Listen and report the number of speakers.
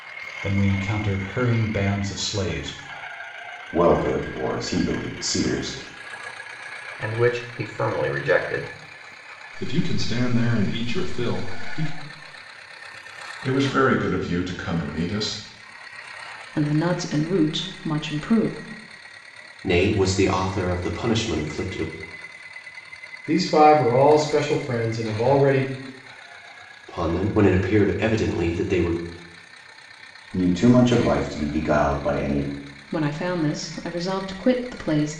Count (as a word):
eight